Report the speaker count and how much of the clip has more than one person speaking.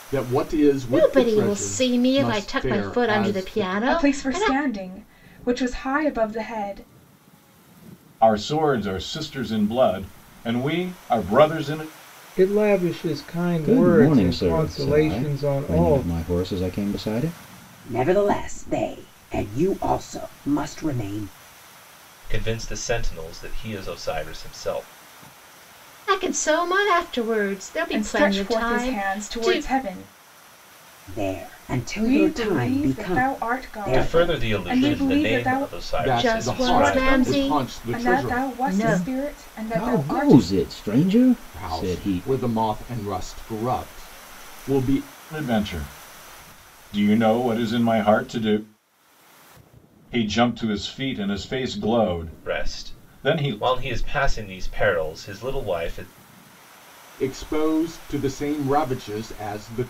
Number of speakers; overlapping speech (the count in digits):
8, about 30%